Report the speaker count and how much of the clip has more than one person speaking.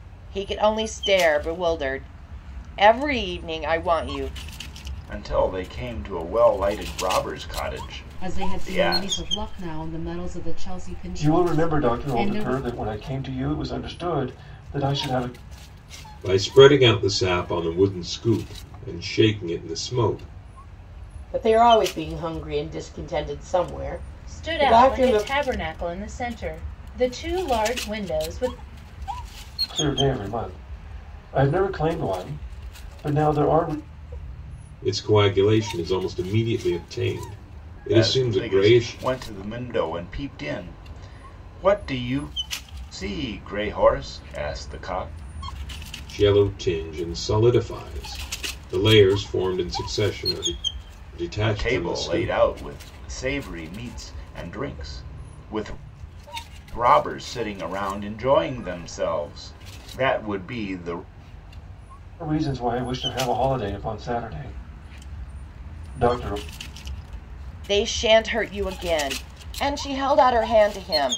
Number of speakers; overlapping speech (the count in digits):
7, about 8%